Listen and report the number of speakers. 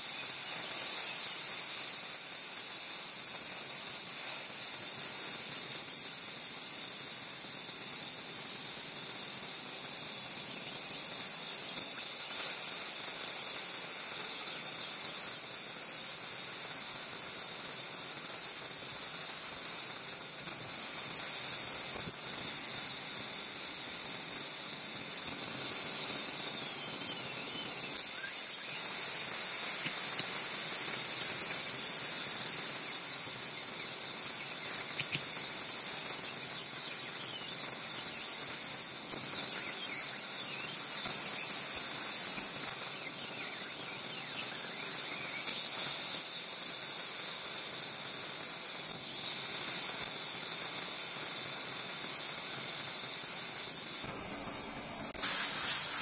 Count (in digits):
0